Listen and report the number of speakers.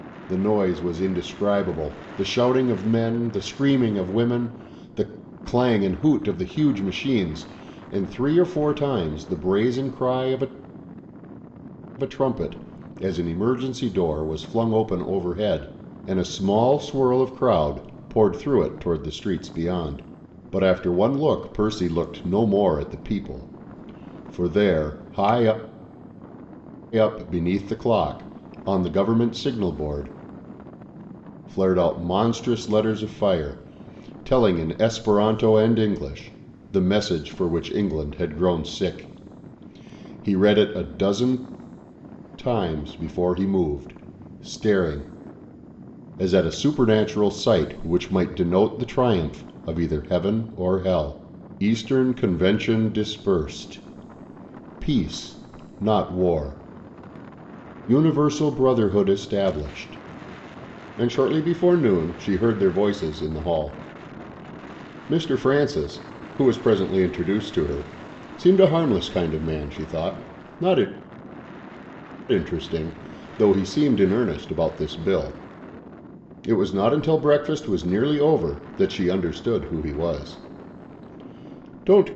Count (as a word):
one